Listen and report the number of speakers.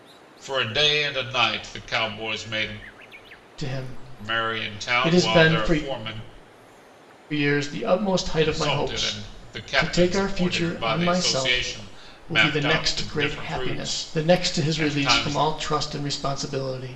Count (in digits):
2